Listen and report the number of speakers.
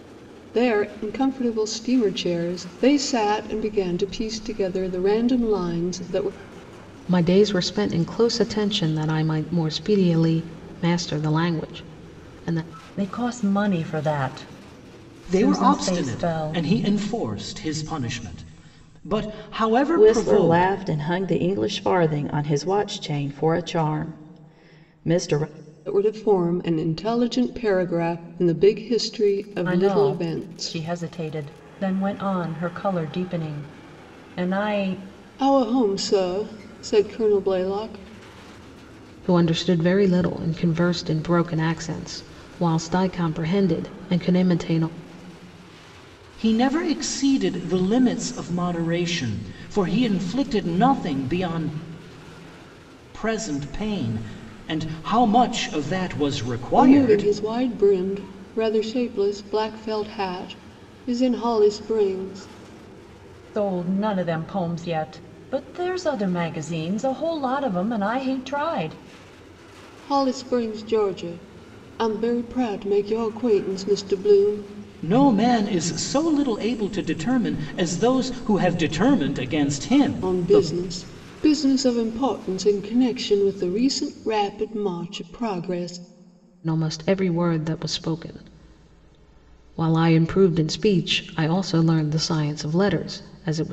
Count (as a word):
five